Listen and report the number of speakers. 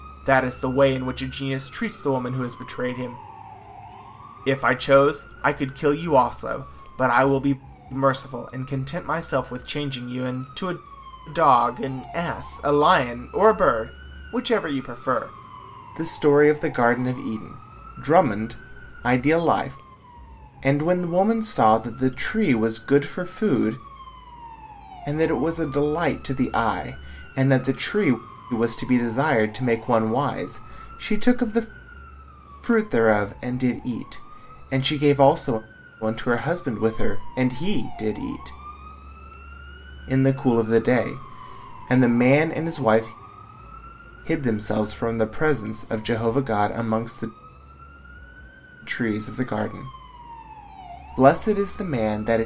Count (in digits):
1